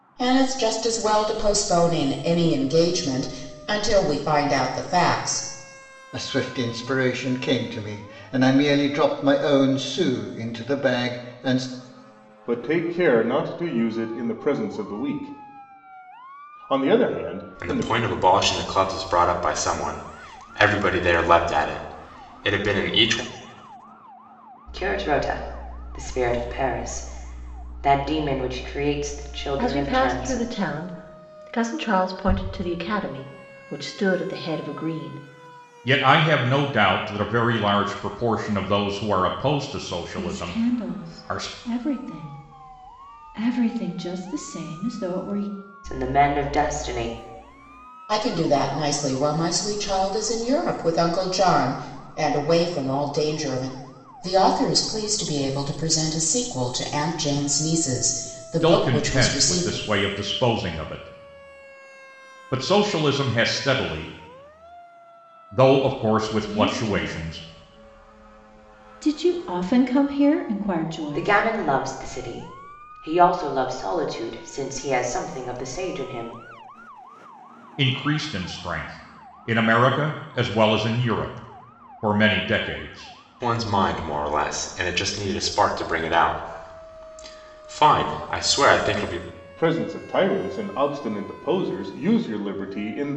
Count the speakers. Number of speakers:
8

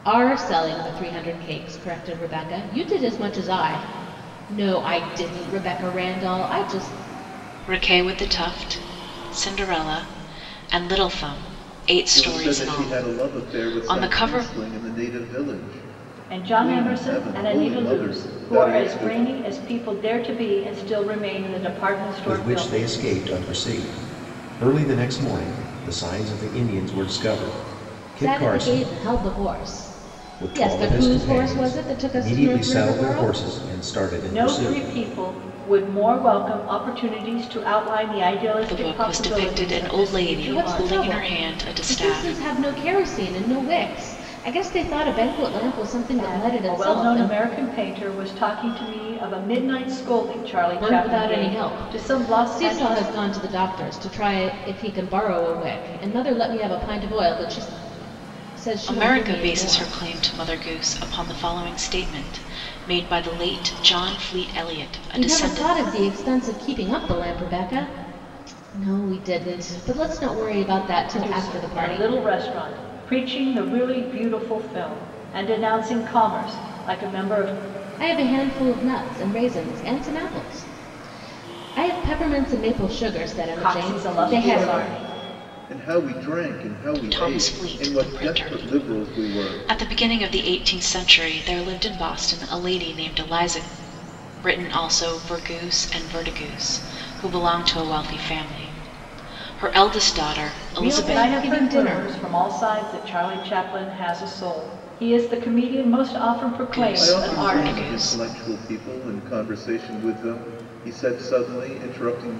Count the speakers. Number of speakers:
5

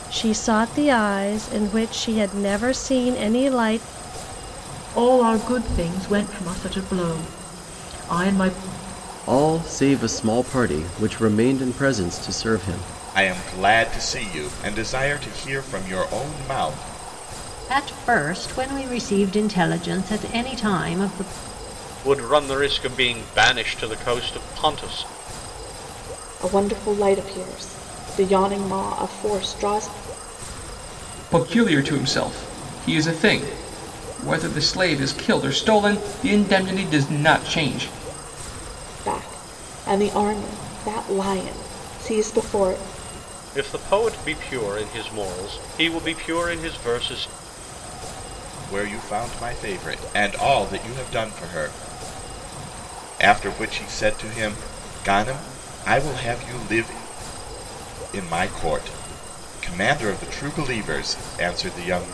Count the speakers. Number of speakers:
8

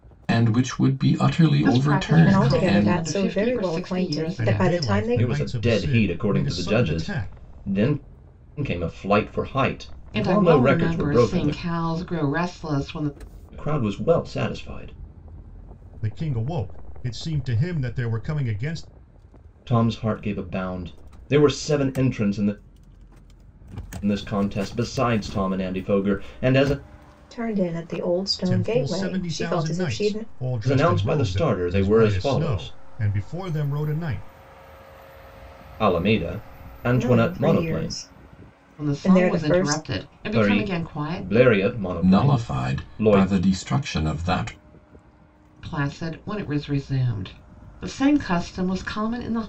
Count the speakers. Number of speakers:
5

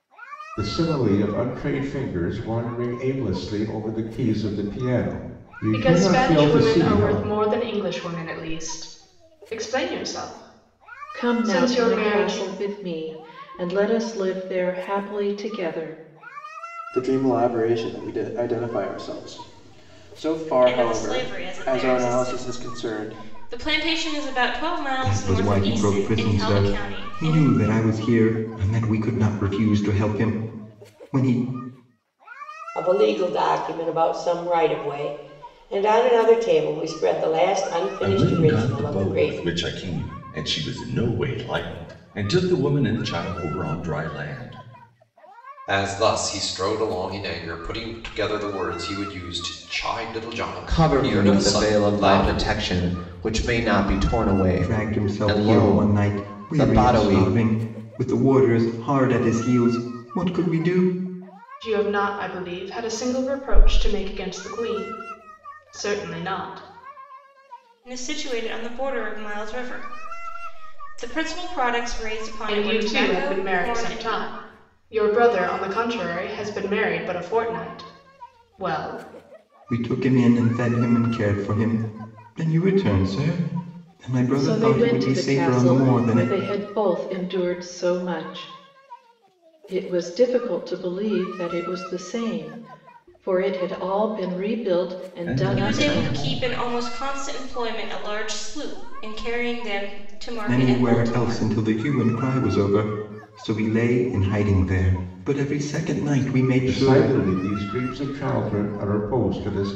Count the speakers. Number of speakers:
10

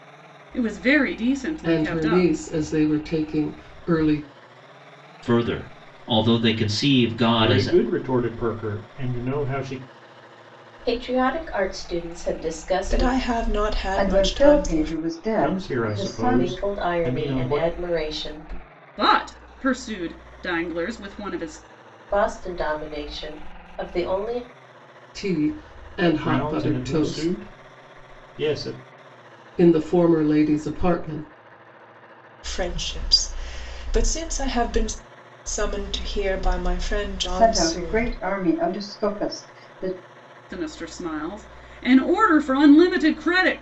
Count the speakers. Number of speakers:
7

